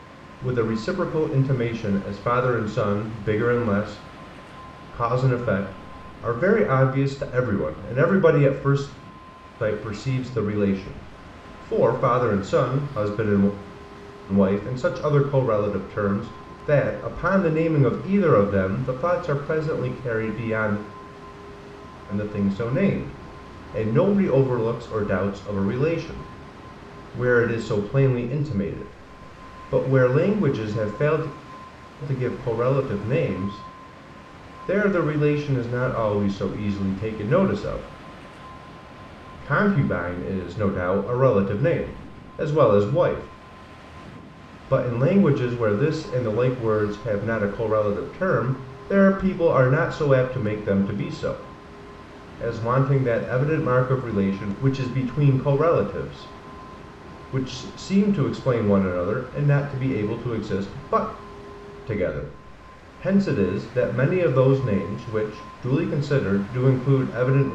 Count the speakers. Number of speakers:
1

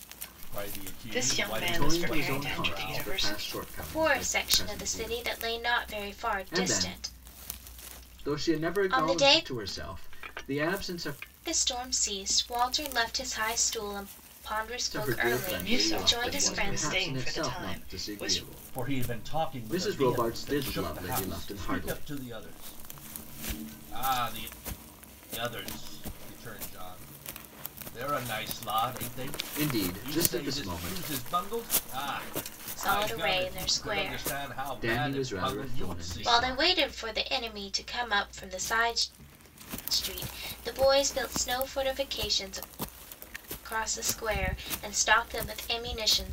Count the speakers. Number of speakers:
4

